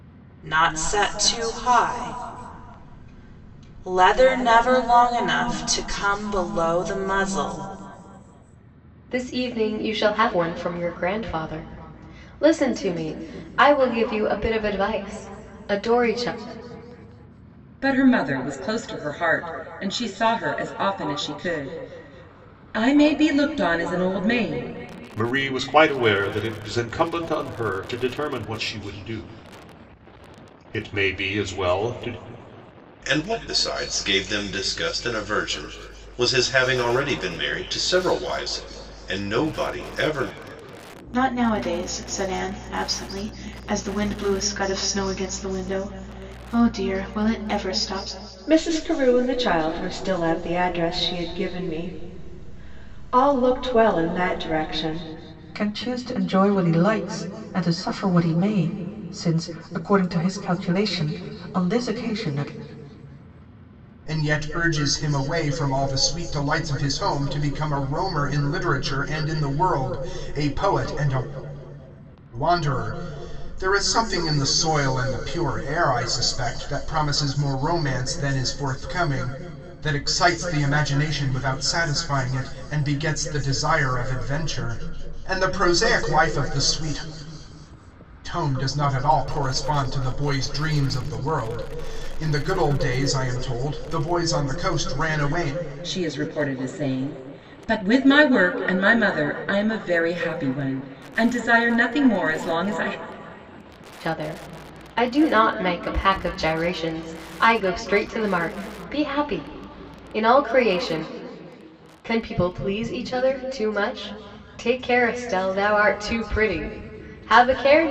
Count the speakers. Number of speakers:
9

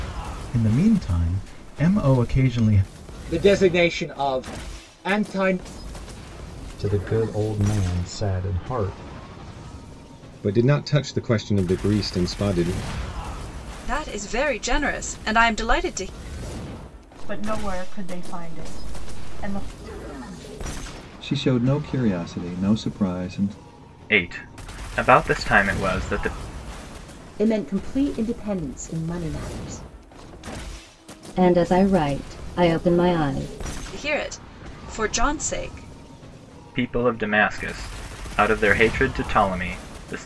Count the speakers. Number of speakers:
10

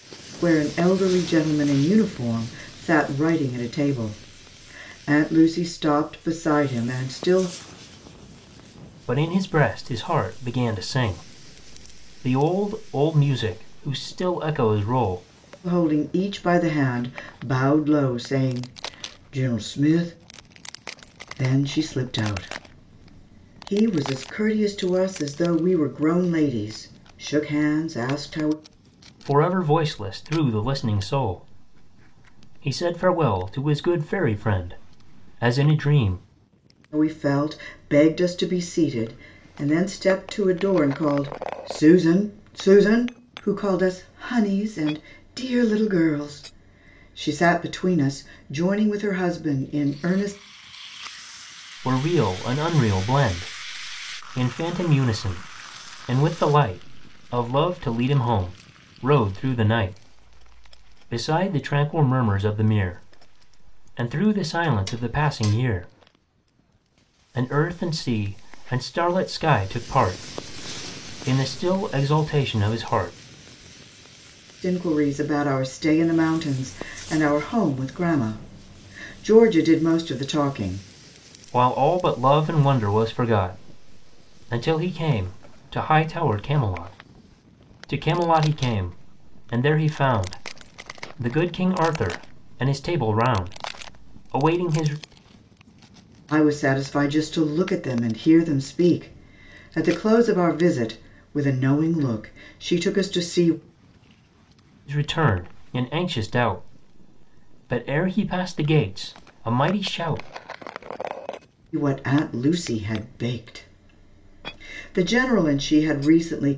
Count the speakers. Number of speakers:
2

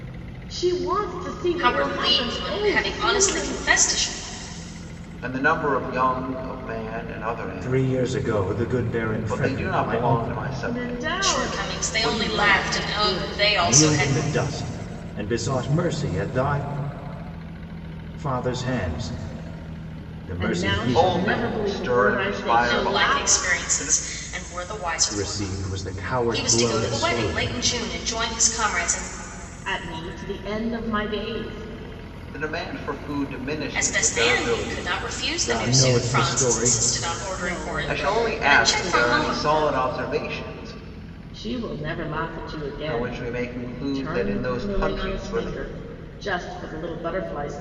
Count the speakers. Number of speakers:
4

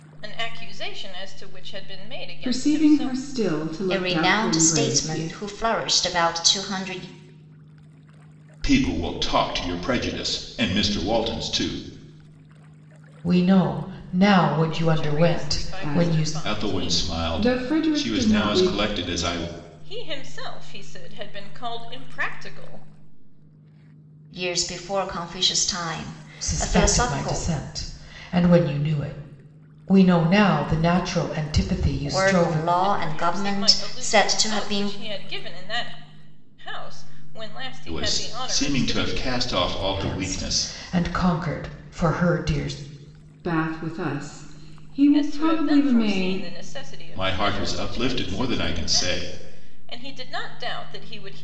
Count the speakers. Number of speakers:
5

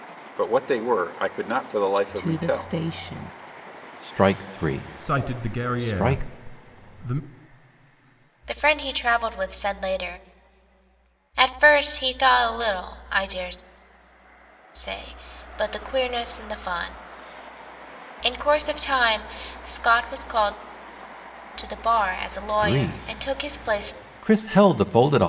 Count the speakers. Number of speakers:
5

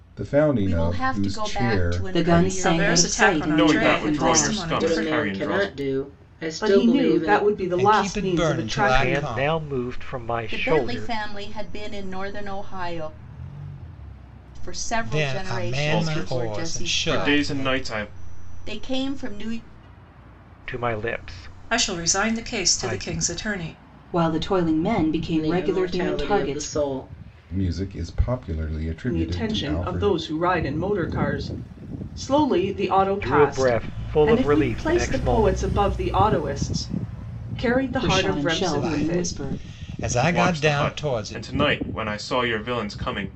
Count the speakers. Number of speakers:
9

